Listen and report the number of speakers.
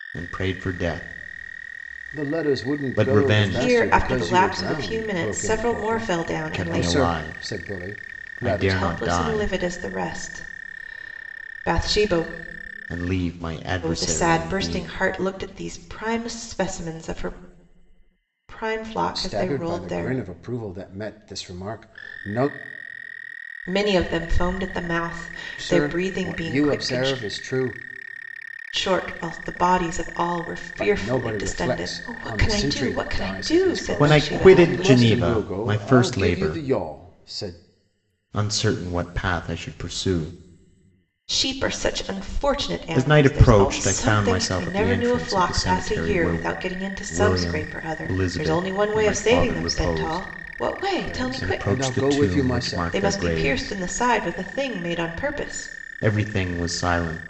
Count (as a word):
three